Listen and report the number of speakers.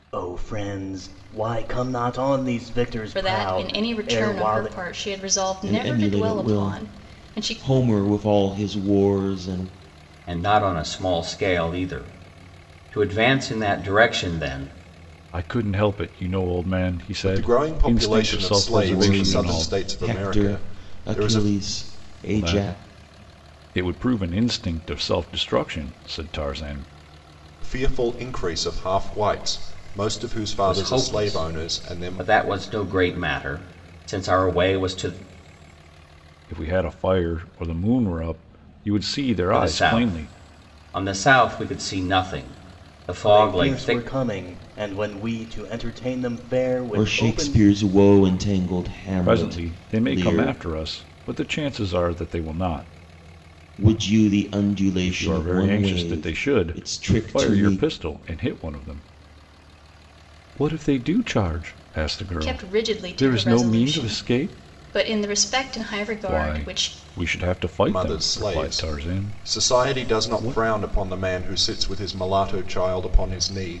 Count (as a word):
six